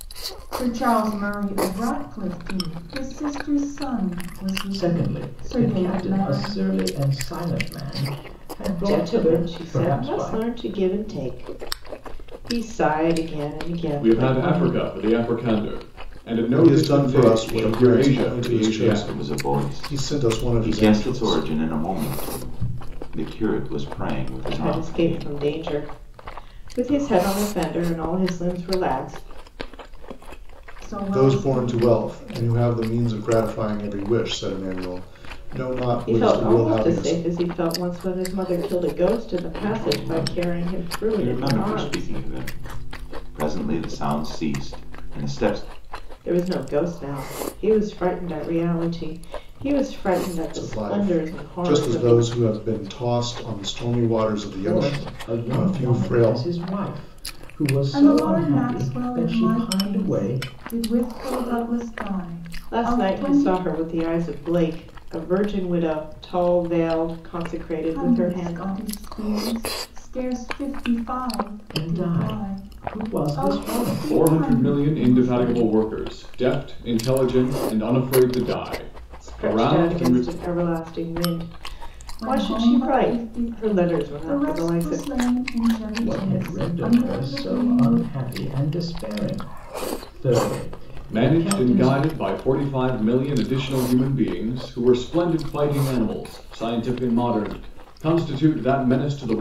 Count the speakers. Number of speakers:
6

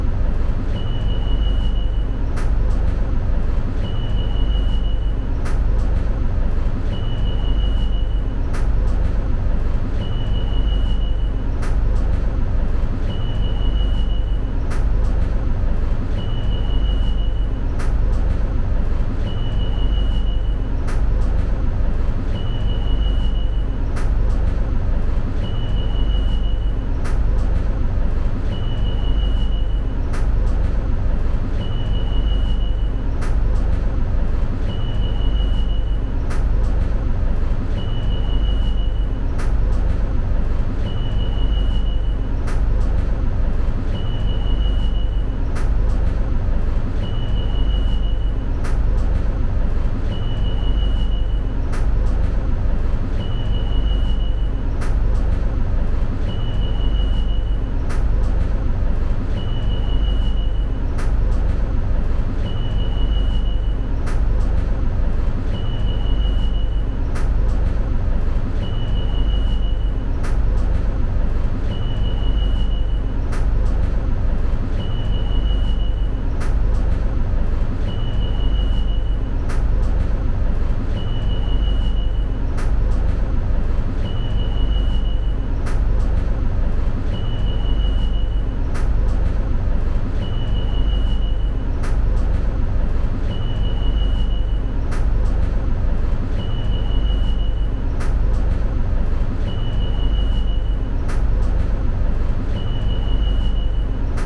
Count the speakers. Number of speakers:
0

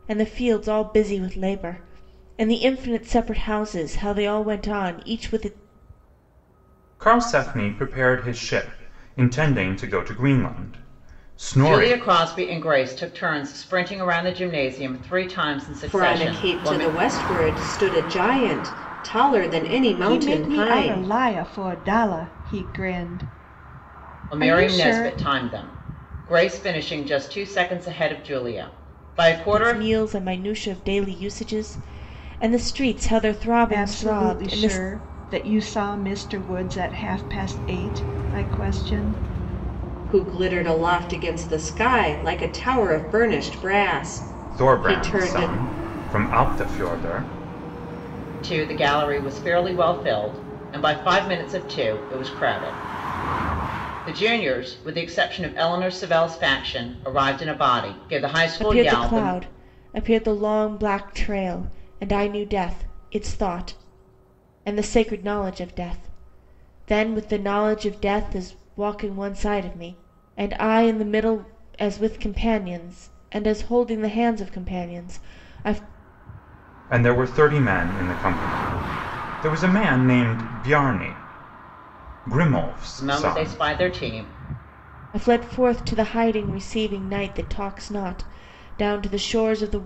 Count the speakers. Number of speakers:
5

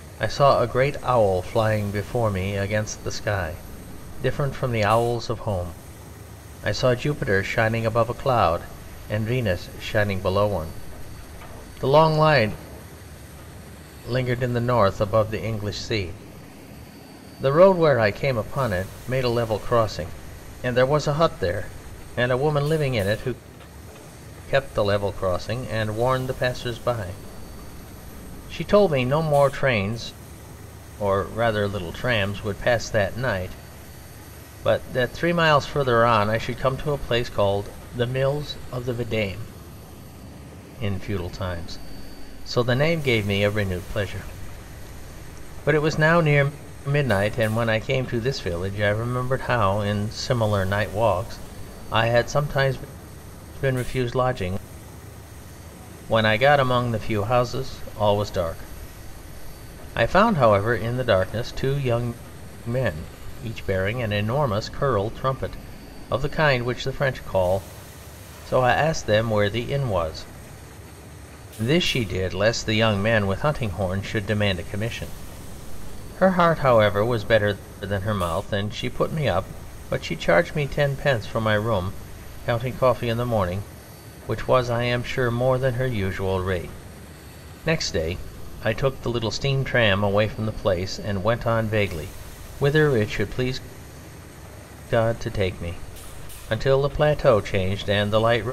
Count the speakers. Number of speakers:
1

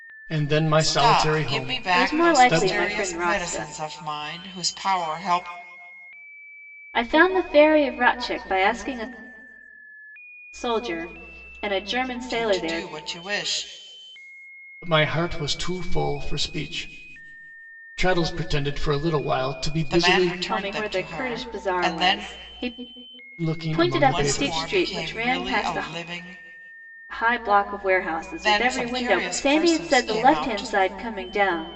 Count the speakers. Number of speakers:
3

